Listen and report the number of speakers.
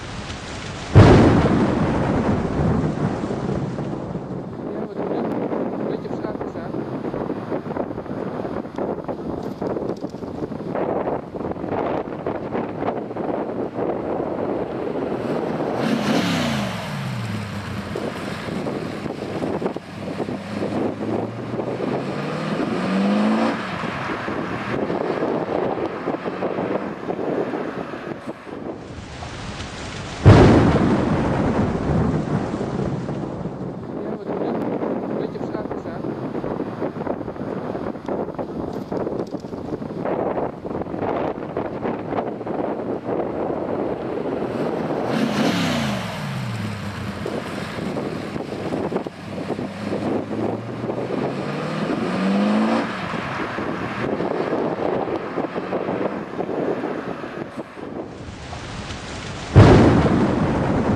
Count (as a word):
zero